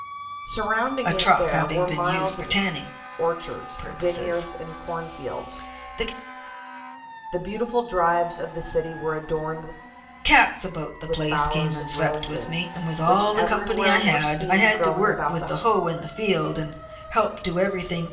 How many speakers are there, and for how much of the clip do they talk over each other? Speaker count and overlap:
2, about 44%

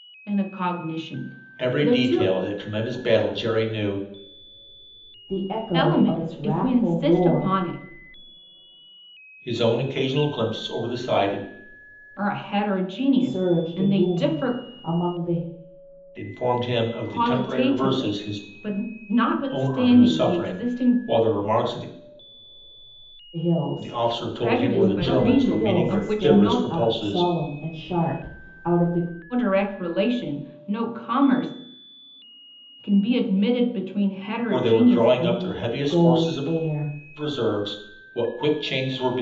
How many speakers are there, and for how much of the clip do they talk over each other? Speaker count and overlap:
3, about 32%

